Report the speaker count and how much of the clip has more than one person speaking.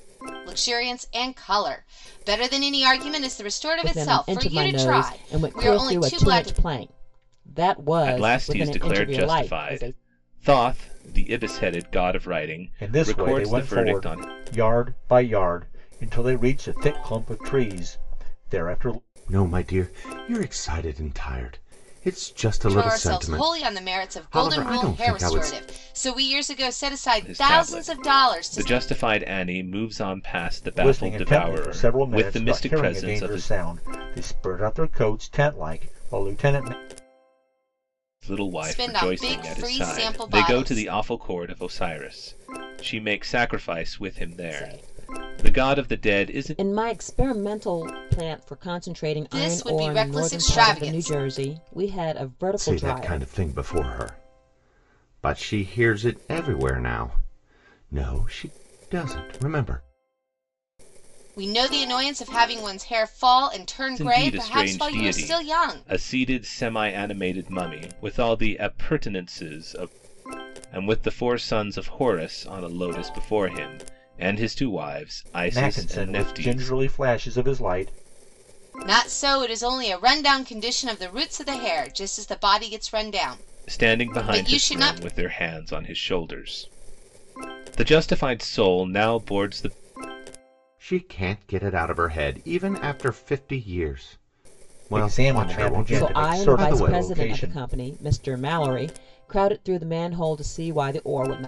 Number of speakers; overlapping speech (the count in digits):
5, about 27%